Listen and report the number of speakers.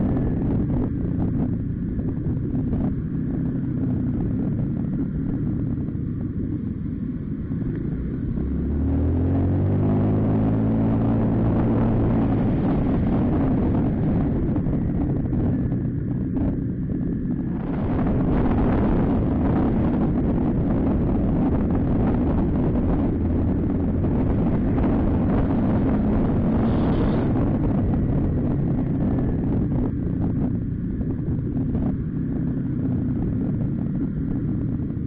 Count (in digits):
0